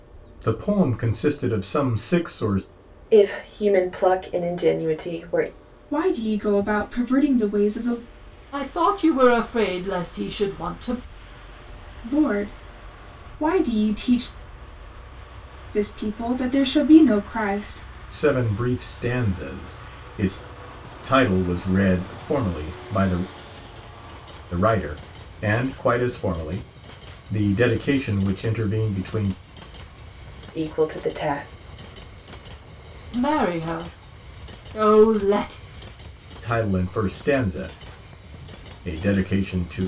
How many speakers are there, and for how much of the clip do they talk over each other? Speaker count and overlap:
4, no overlap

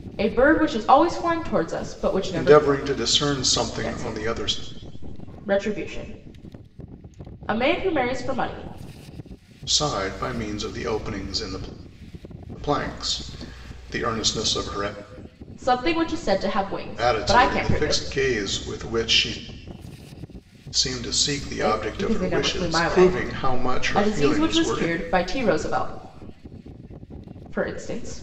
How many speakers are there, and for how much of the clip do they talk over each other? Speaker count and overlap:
2, about 17%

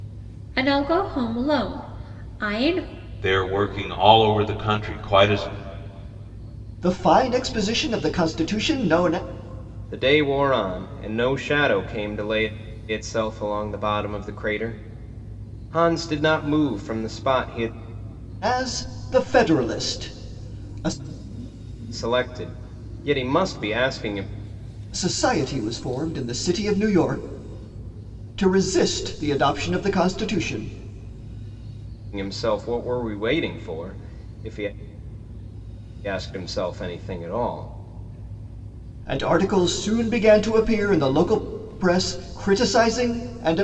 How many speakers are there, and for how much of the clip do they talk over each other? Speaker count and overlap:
4, no overlap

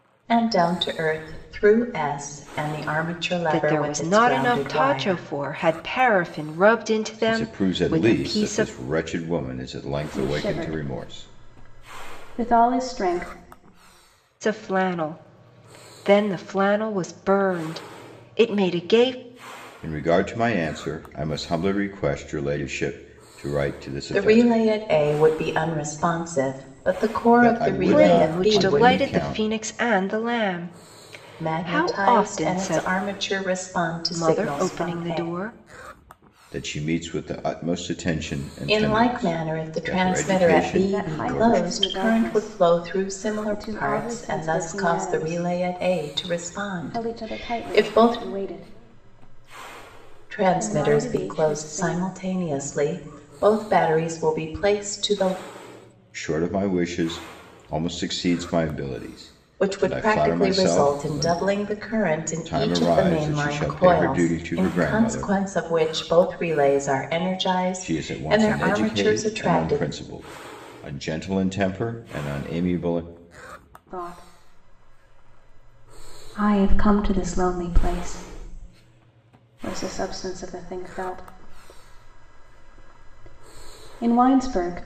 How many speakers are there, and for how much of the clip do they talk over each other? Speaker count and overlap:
4, about 32%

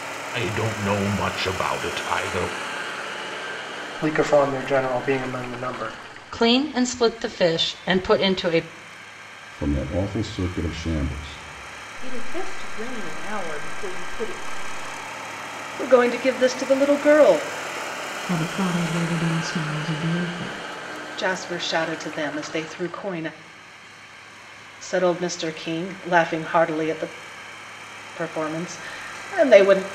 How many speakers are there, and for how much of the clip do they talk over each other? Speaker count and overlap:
7, no overlap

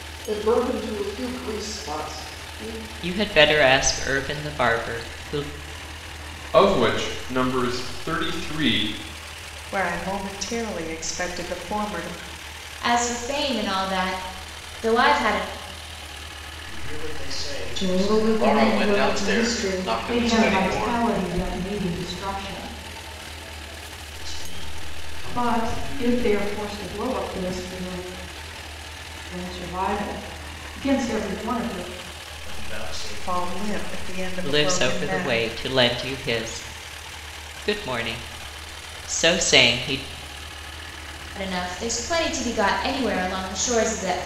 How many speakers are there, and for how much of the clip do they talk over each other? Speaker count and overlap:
9, about 15%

